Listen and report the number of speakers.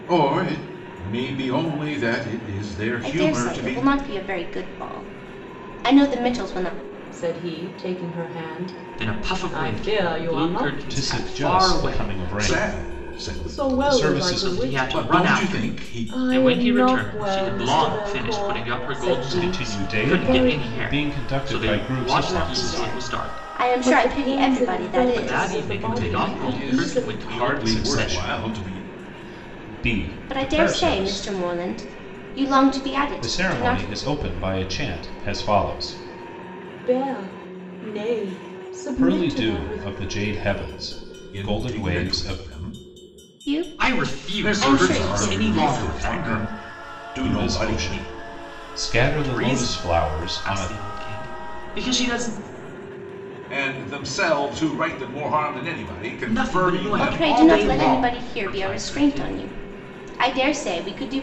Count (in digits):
5